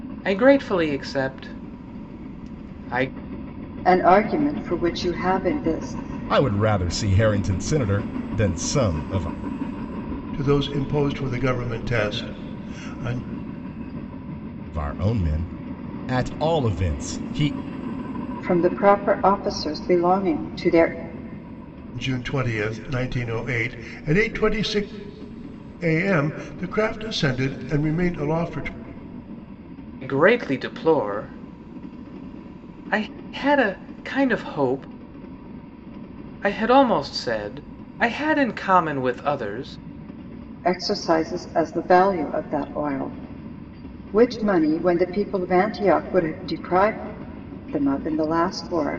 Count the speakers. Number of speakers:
4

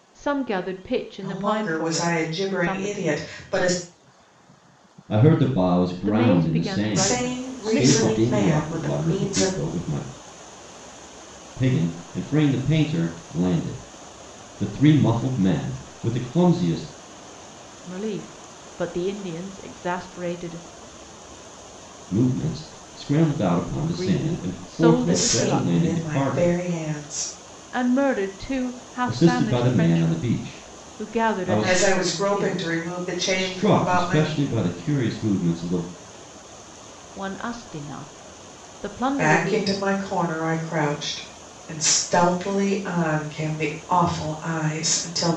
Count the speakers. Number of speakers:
3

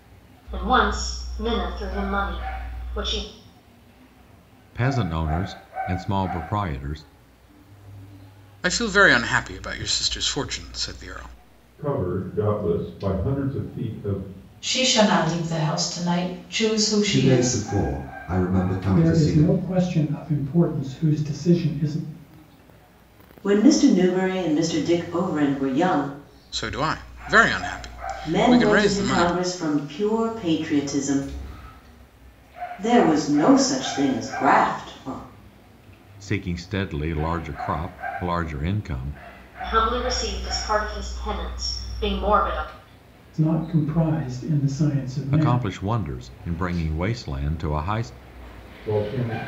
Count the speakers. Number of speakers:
8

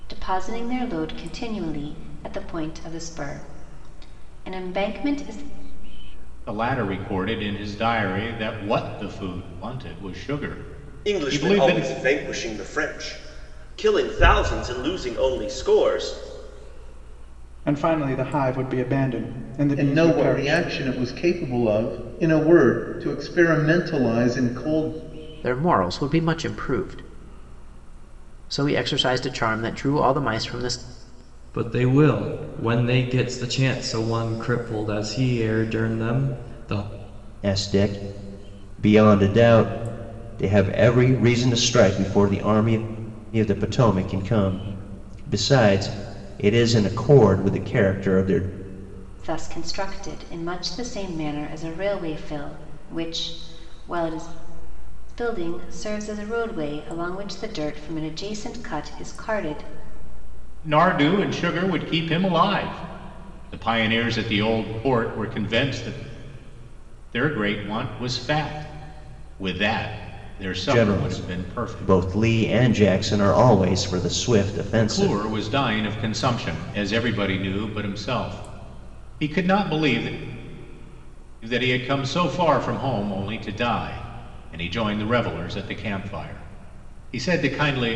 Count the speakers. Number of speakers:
8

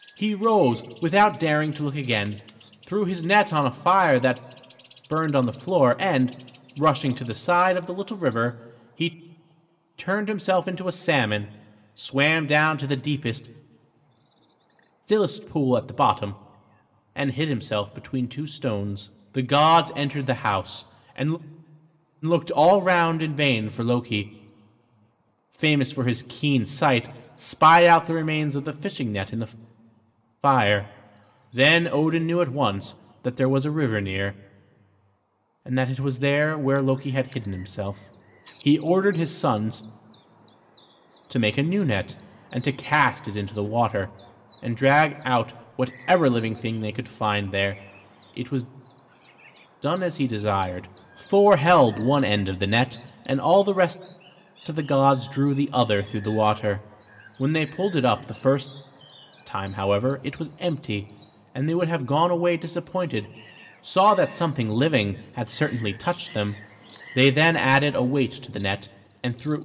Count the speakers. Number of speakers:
1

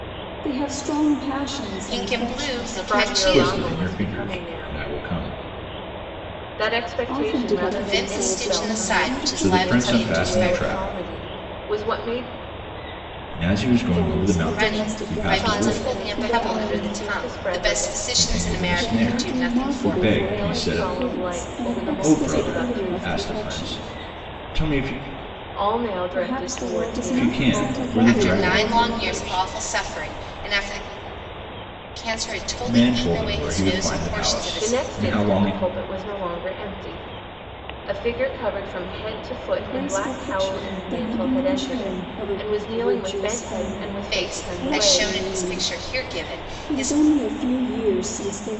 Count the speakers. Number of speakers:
4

